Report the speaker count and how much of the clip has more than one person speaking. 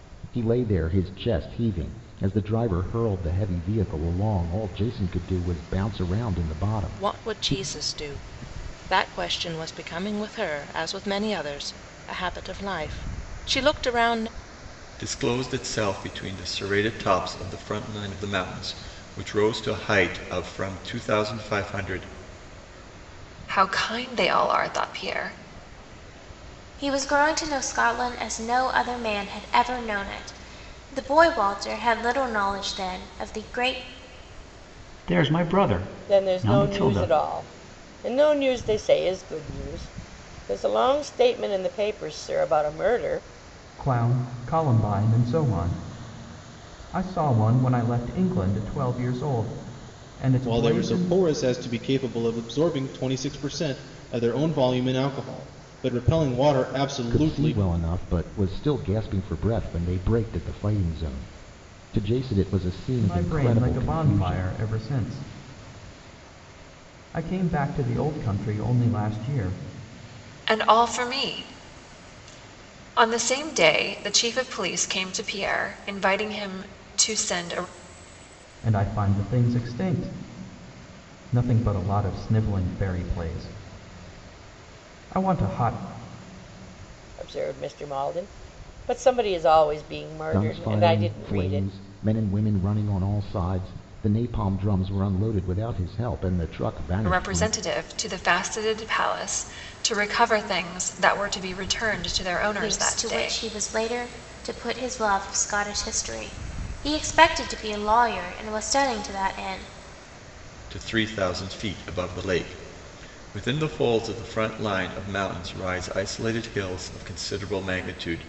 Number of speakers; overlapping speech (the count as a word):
nine, about 6%